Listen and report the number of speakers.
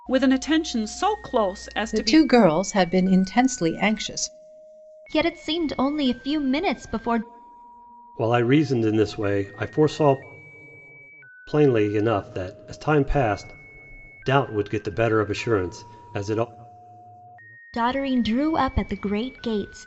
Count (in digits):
4